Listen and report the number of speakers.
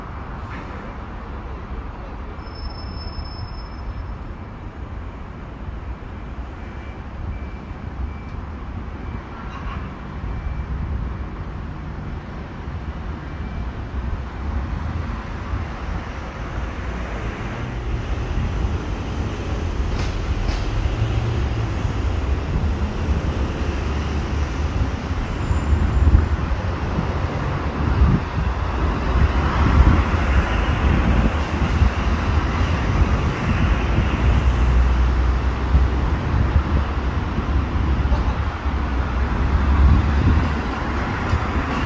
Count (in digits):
0